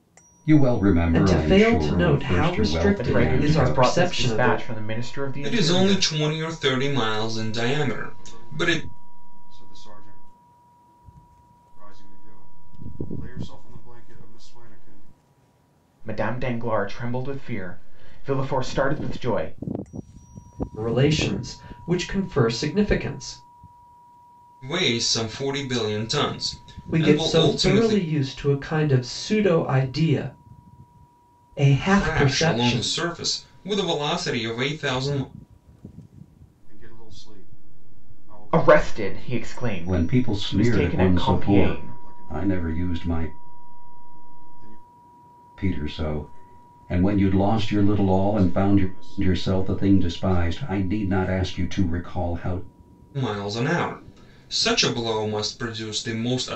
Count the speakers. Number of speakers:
5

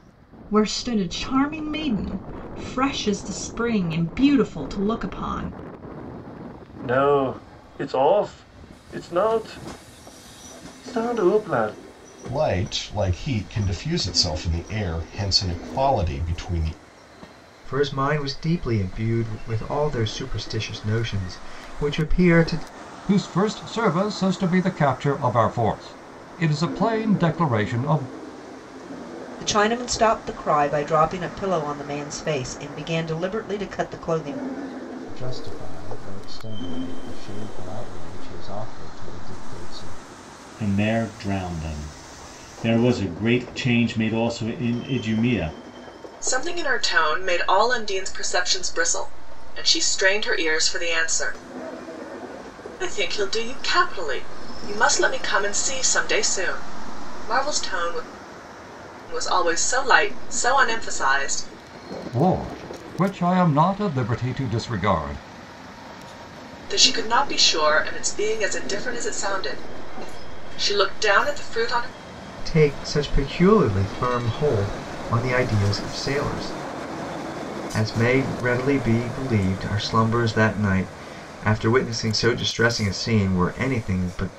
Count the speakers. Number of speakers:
9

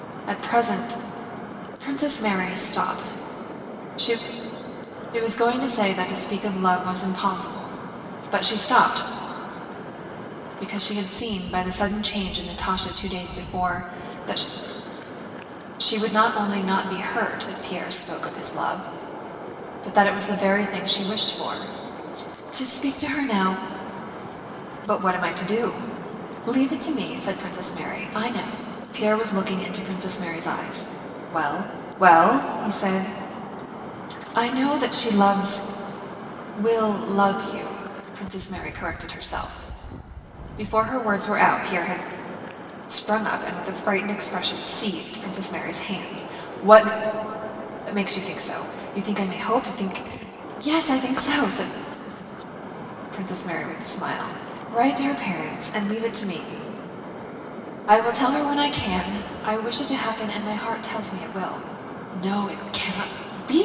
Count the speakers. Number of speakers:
1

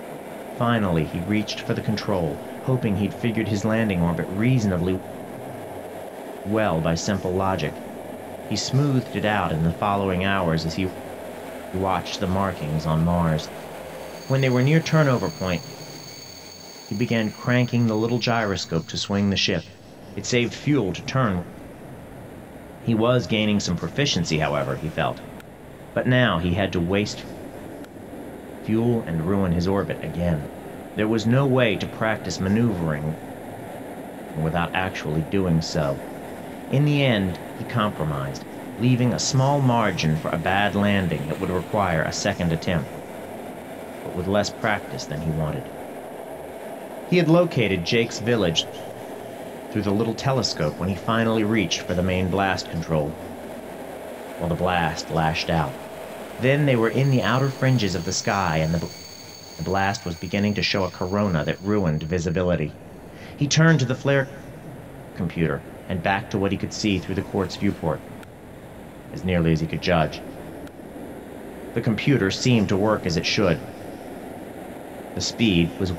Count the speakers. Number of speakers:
1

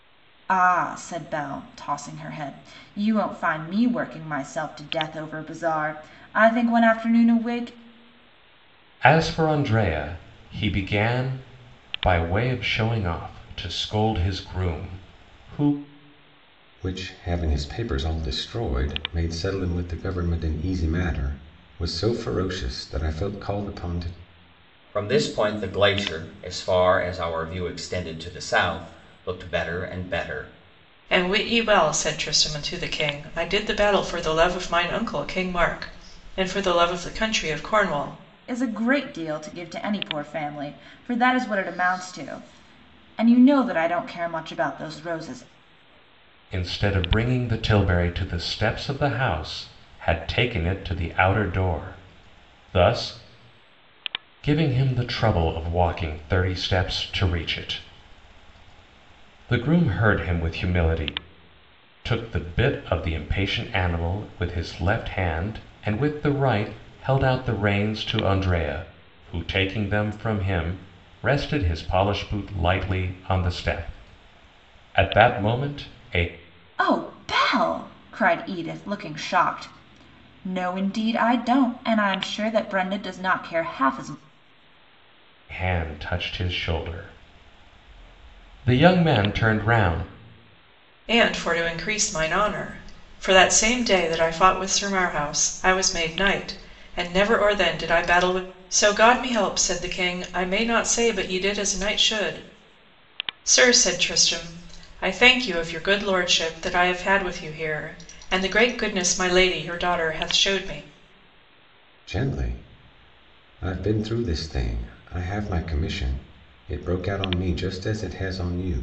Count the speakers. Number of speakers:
5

